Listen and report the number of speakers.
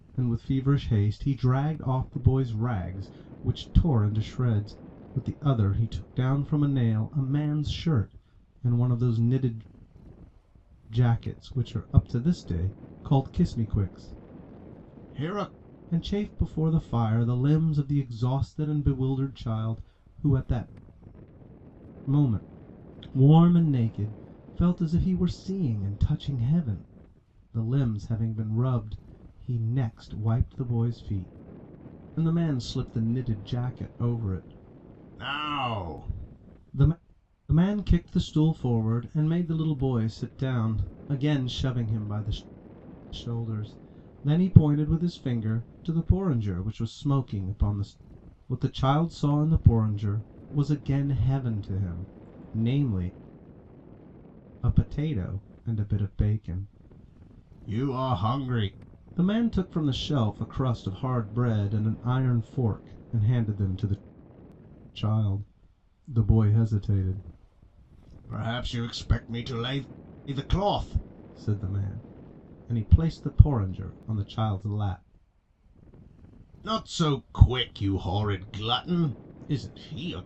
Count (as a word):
one